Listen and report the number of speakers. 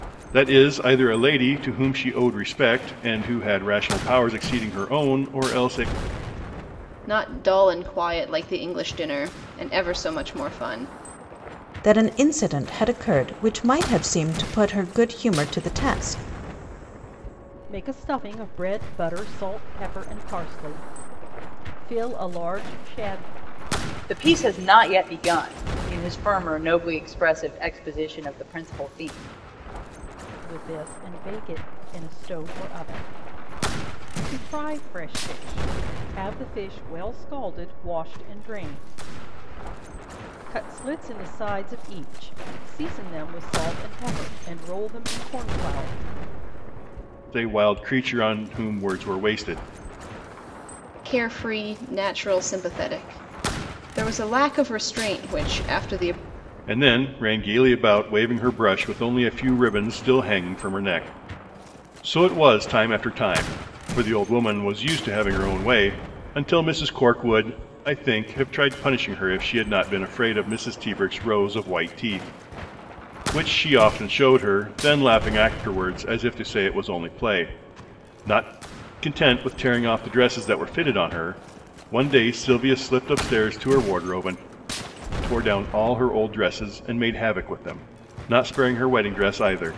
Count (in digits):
5